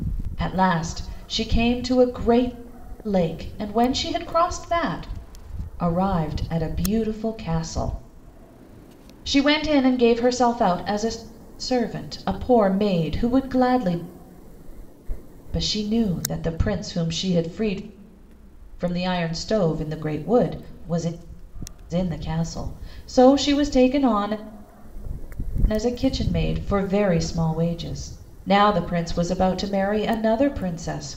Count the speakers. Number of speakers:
1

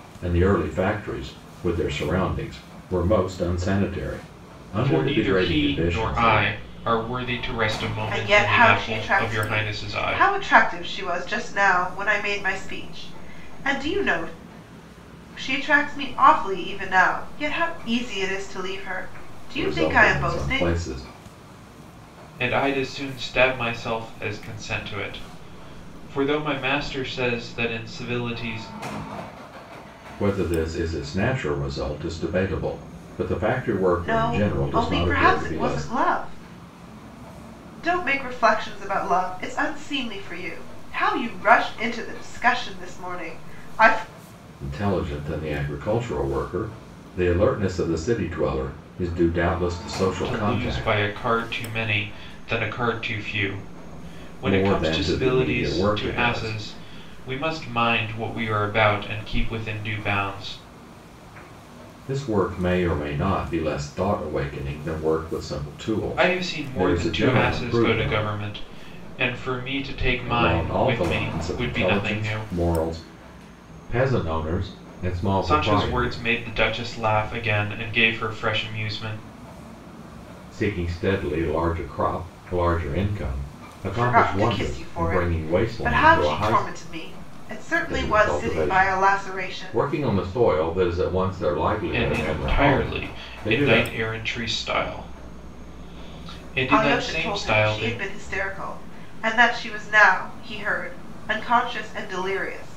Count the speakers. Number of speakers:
3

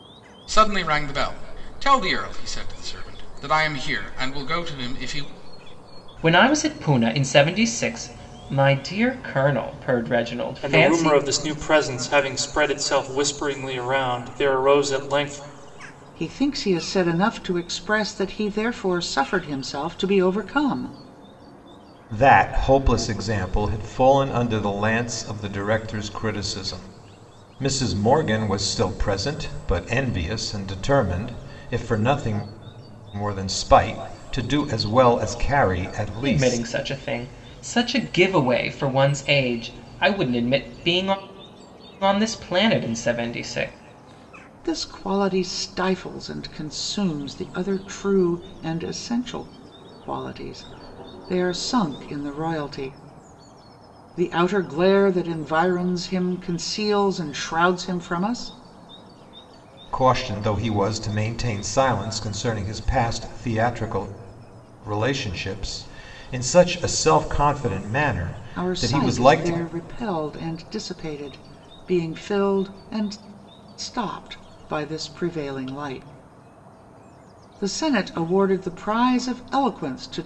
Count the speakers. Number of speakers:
5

